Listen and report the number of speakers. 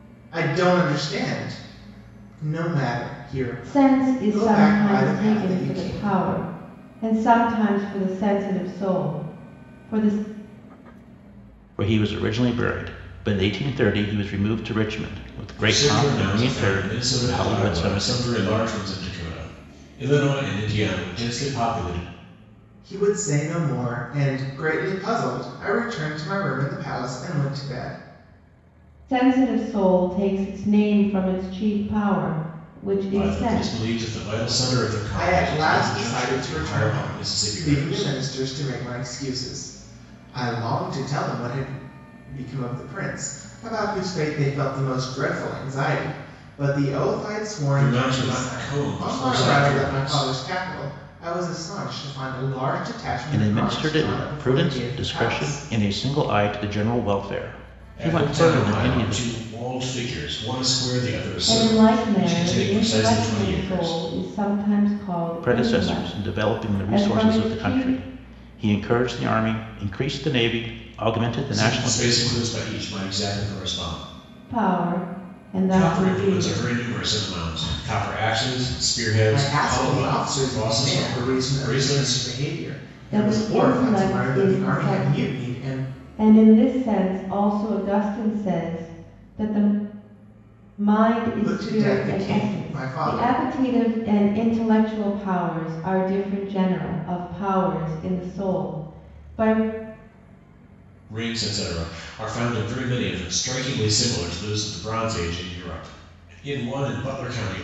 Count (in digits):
4